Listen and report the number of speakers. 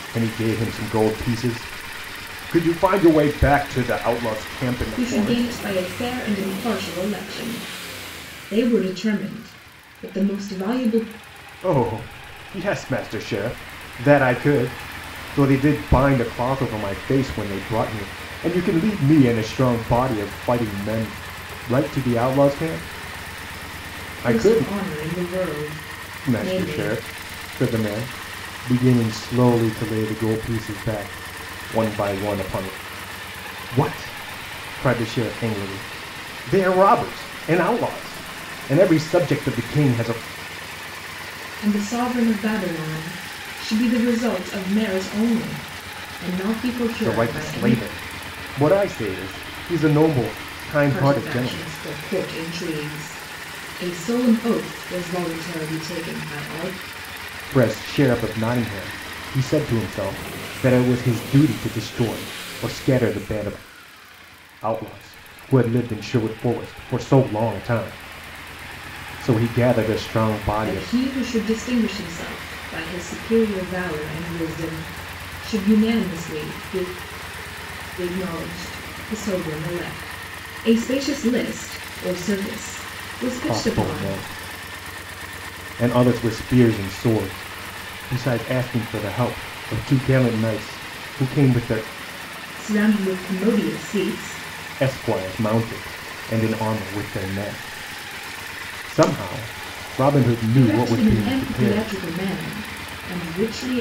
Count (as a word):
two